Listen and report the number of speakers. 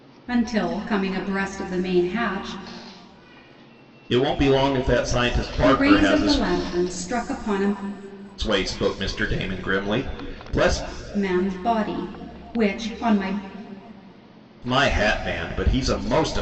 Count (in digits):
2